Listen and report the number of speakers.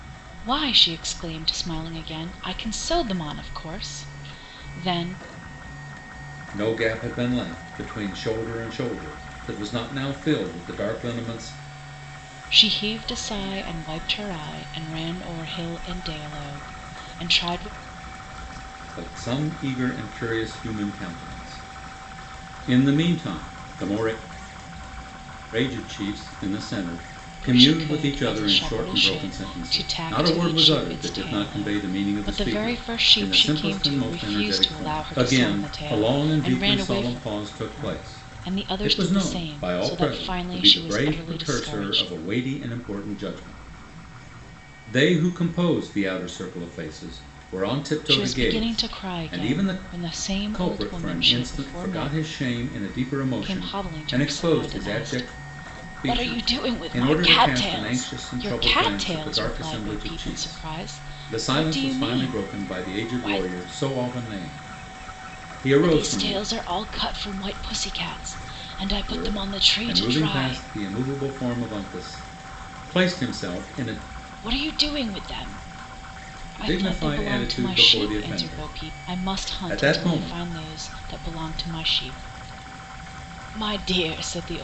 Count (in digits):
2